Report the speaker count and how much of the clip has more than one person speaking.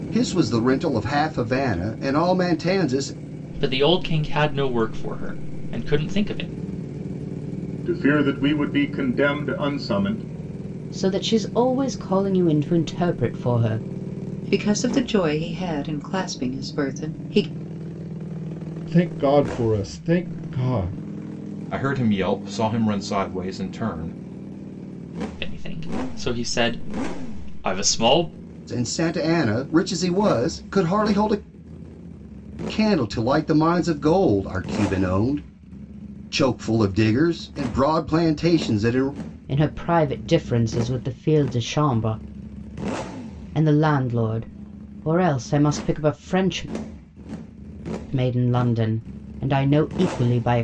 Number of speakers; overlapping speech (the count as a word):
seven, no overlap